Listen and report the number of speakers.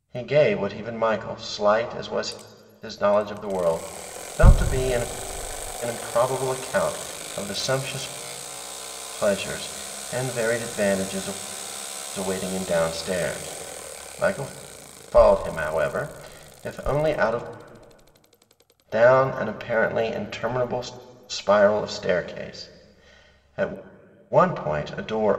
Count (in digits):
1